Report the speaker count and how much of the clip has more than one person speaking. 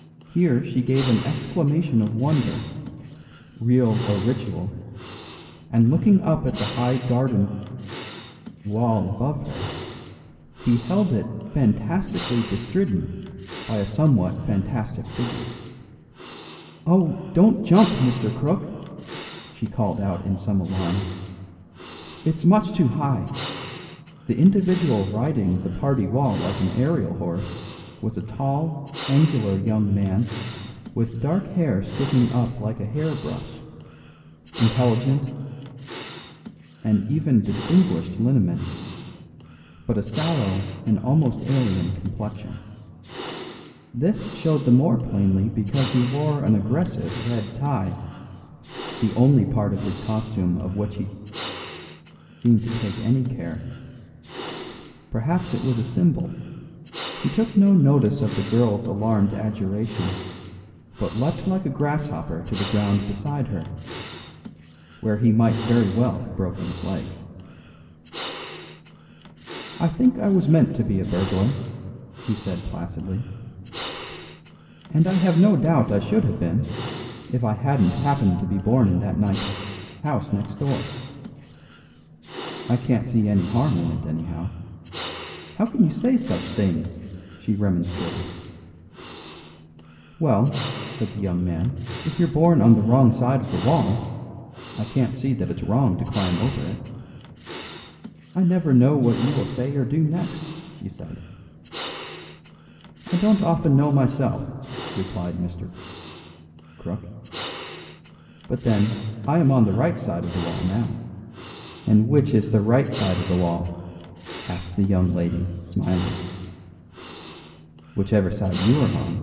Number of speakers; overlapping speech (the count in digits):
1, no overlap